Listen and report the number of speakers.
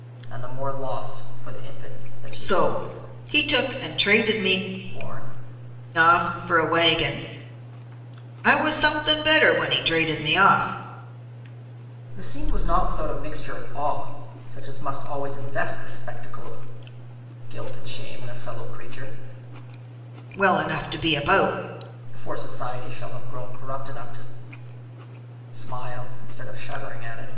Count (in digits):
2